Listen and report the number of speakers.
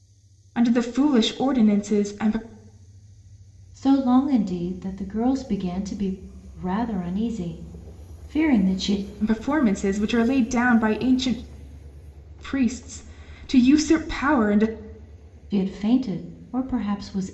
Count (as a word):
two